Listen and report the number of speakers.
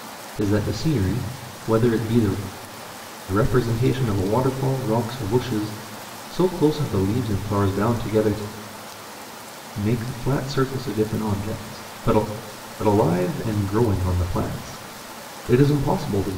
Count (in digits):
1